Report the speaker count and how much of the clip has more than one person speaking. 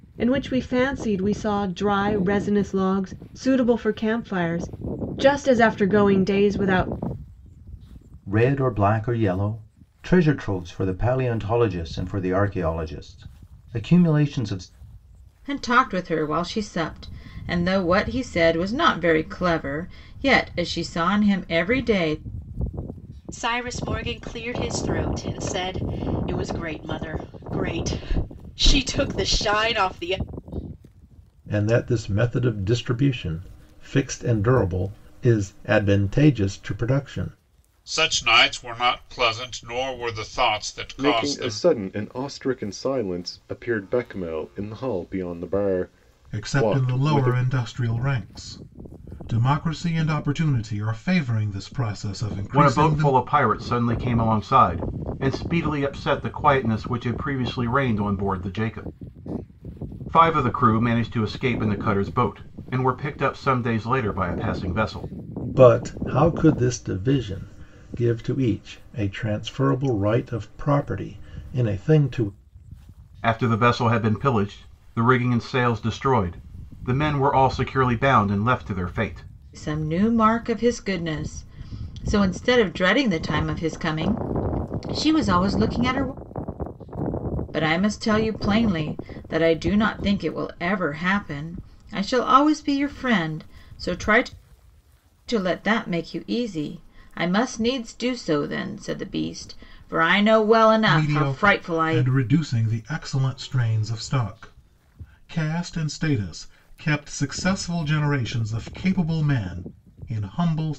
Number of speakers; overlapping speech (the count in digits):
9, about 3%